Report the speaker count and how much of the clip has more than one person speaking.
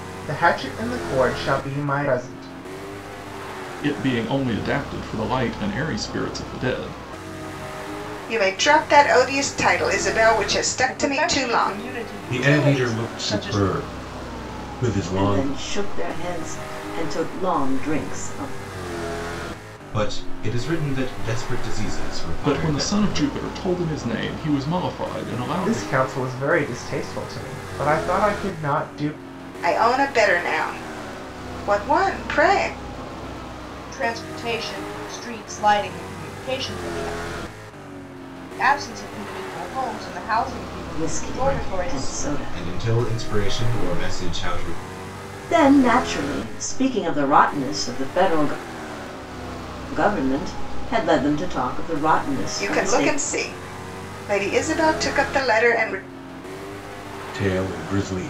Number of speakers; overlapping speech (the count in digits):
7, about 11%